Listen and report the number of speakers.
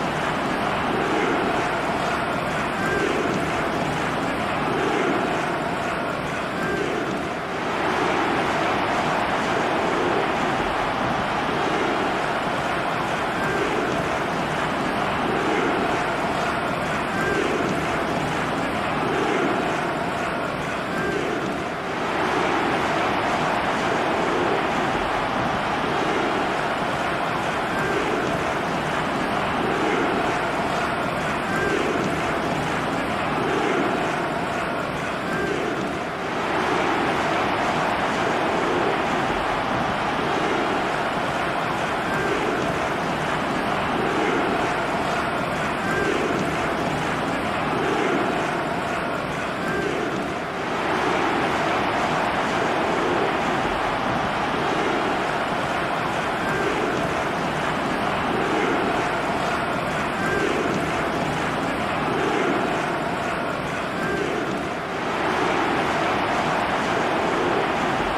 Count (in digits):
0